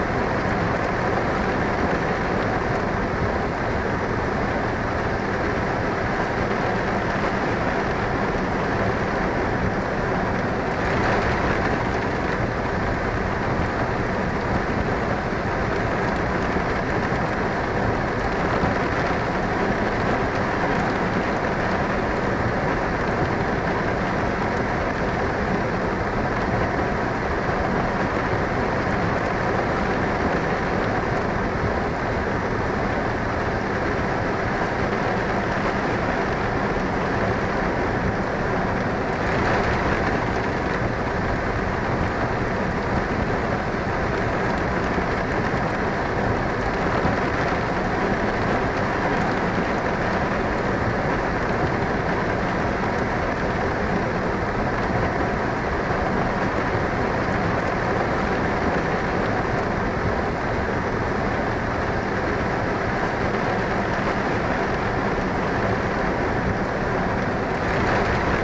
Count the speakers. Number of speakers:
0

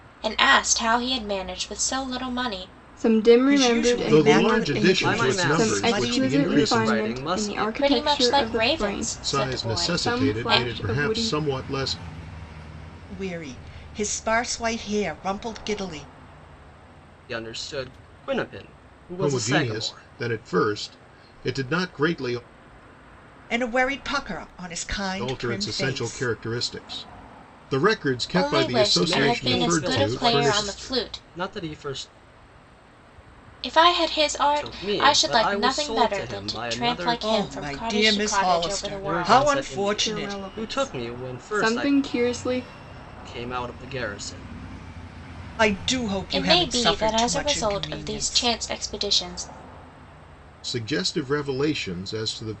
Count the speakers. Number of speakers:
5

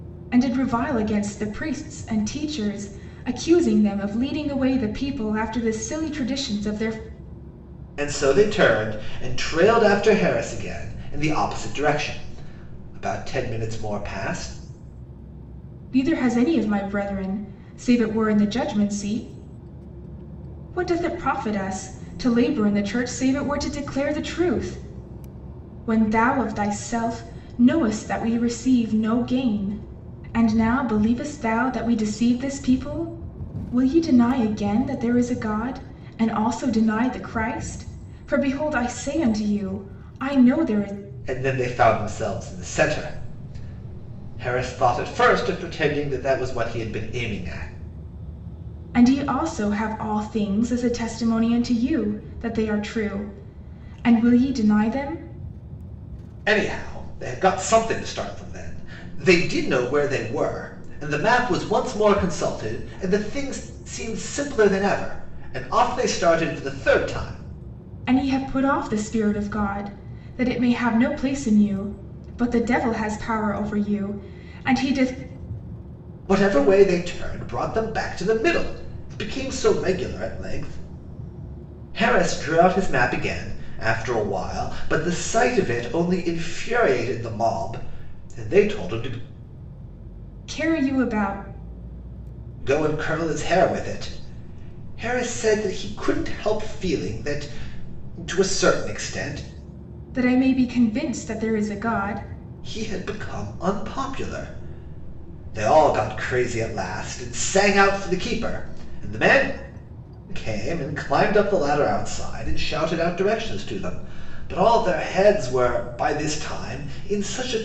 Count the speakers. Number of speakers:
2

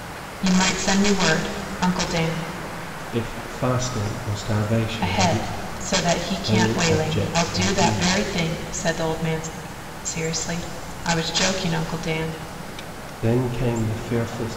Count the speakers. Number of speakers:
2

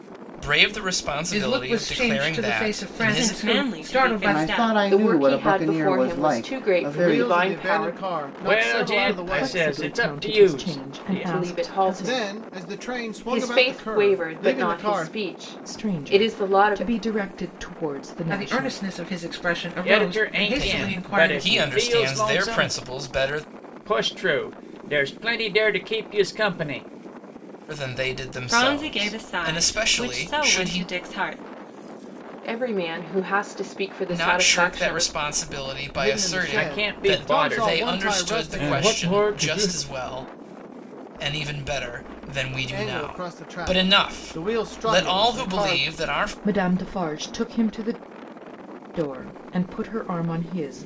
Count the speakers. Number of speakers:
8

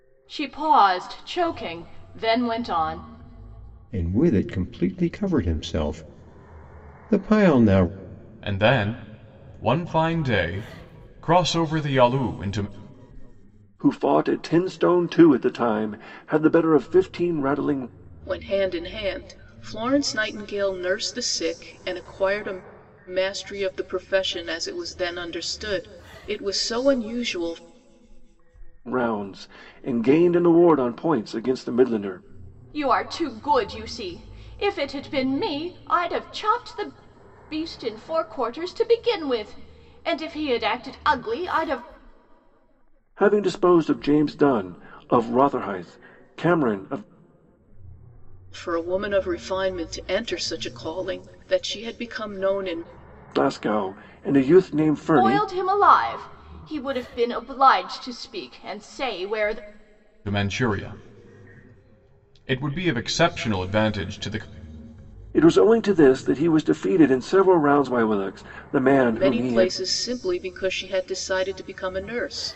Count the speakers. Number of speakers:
5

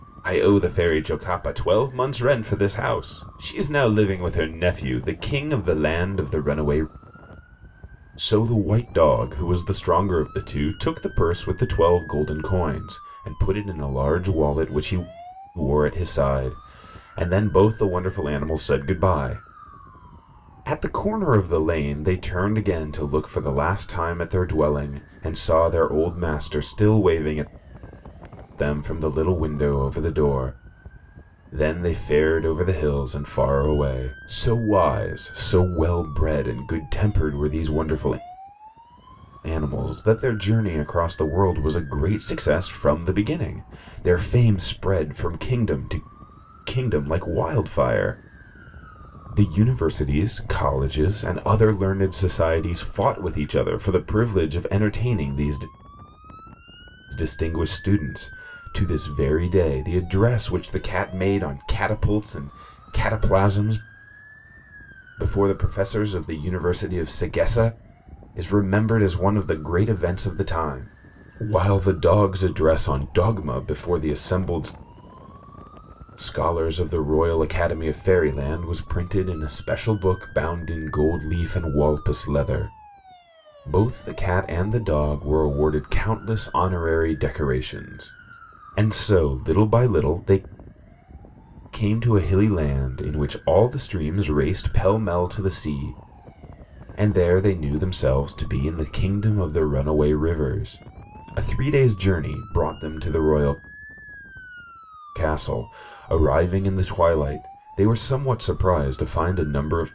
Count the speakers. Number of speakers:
1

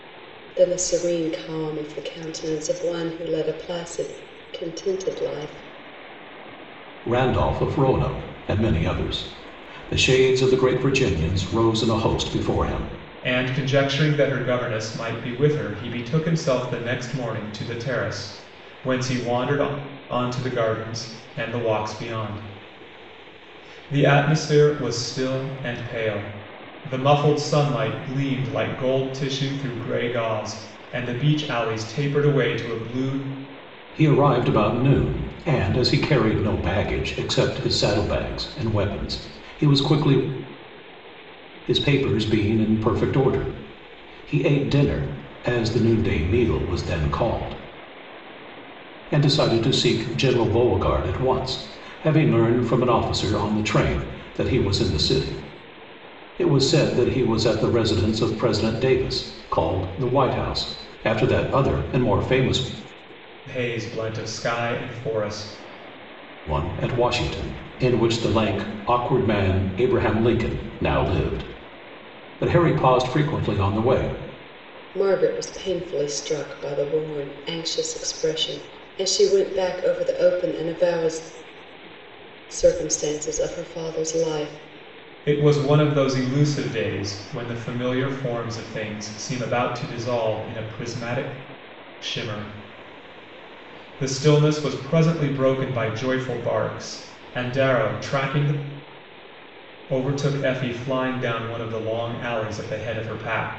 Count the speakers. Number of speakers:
3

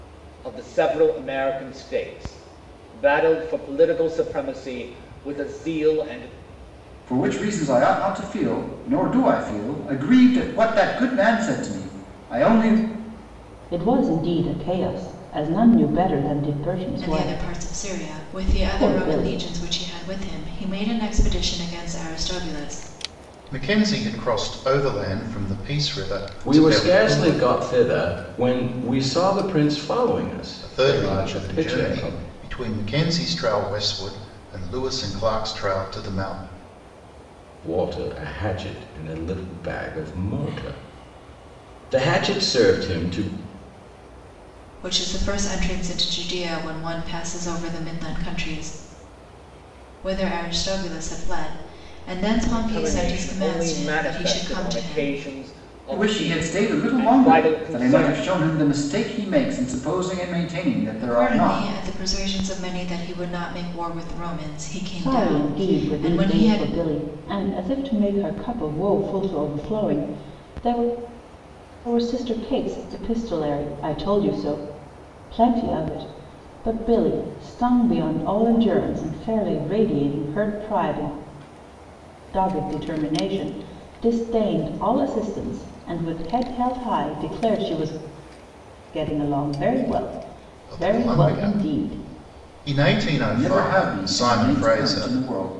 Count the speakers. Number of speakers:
6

